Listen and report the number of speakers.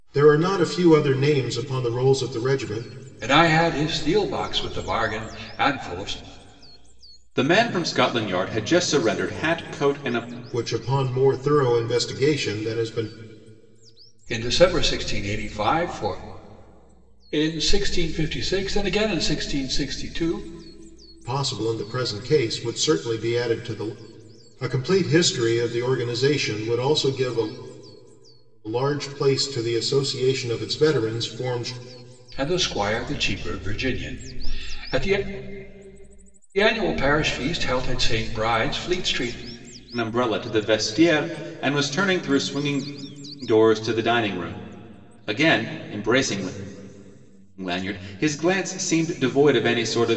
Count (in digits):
3